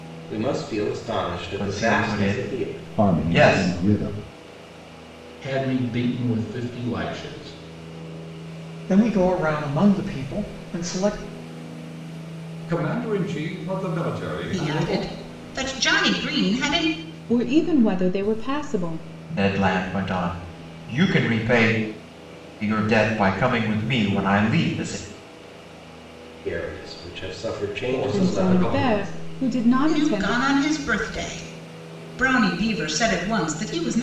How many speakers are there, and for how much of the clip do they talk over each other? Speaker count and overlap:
8, about 13%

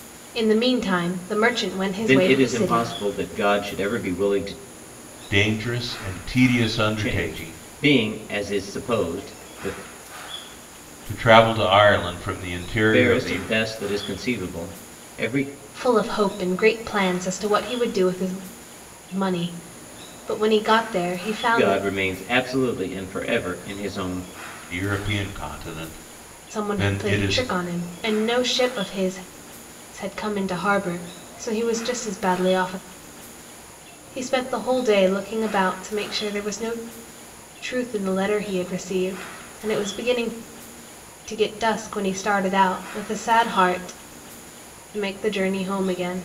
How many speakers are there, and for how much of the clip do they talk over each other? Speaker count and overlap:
3, about 8%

